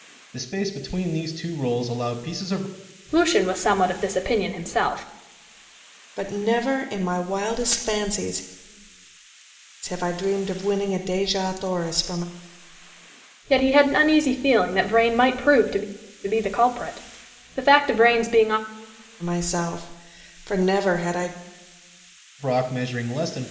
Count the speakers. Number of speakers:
three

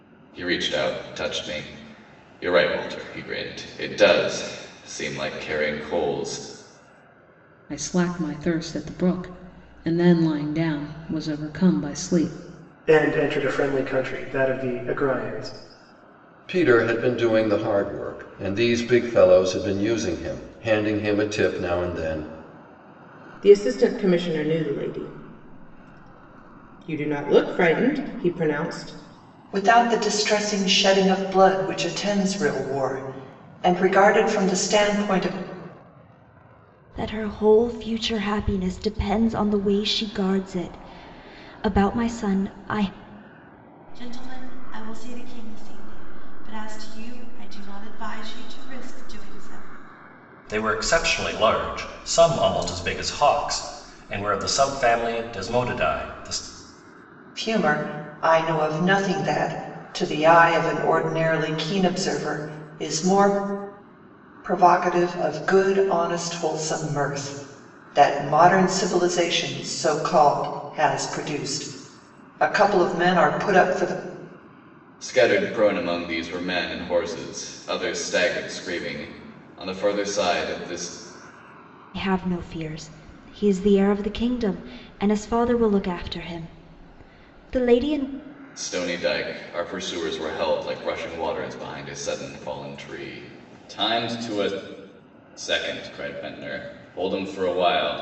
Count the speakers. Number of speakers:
nine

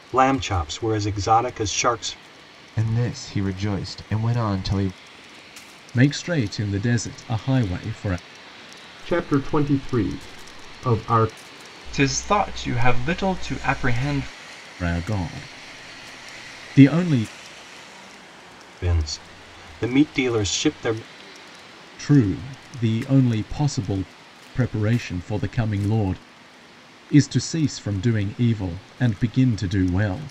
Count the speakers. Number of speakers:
five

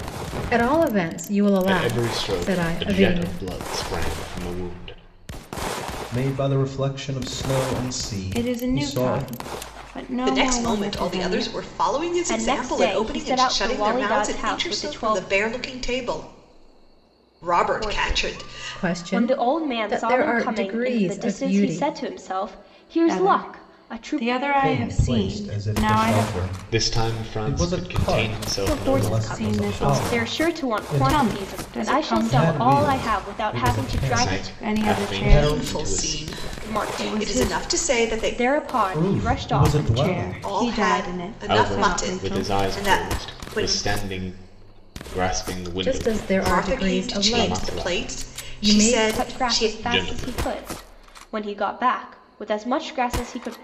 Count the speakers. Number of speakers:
six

